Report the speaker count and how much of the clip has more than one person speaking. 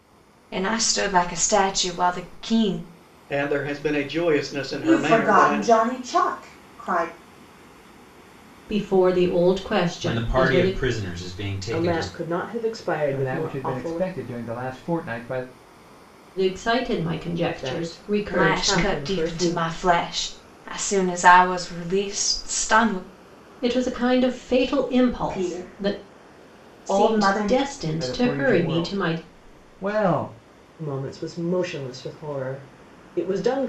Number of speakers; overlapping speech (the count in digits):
7, about 24%